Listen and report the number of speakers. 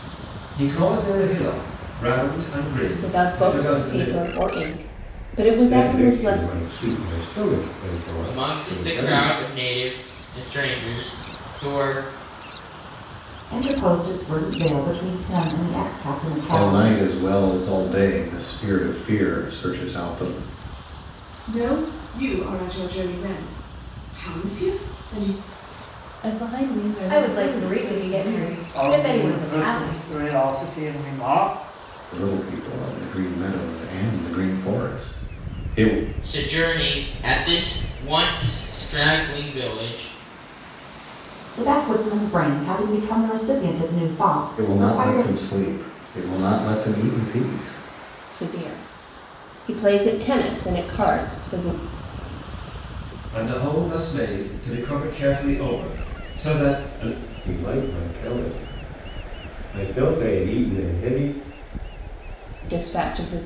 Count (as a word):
ten